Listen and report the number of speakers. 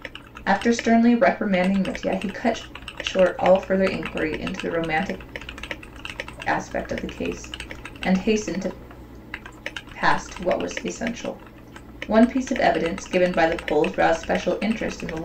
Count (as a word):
one